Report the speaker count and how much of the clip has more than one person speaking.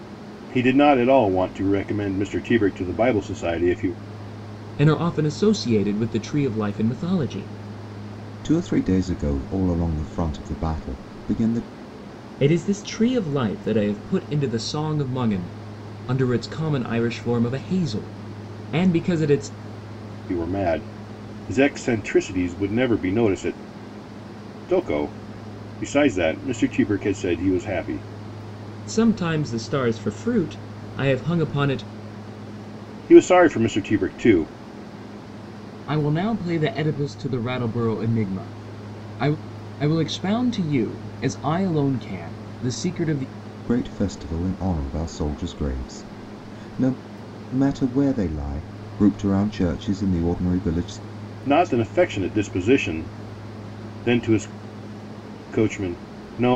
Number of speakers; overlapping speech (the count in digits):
3, no overlap